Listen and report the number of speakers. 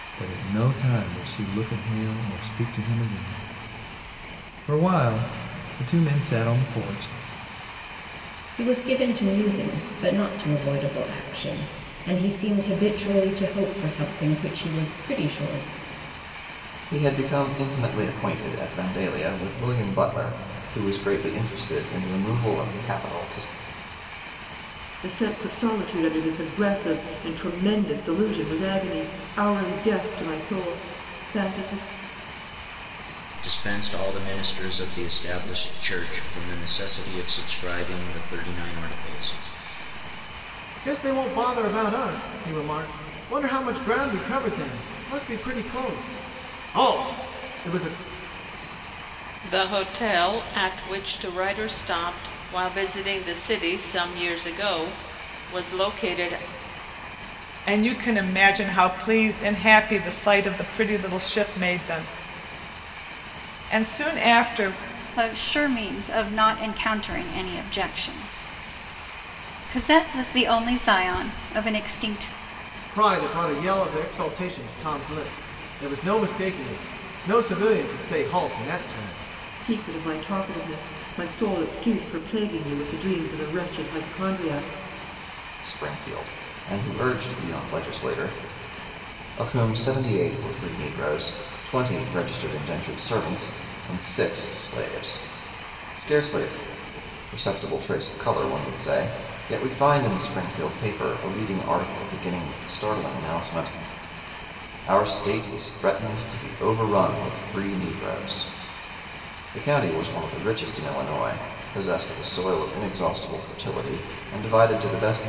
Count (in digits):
9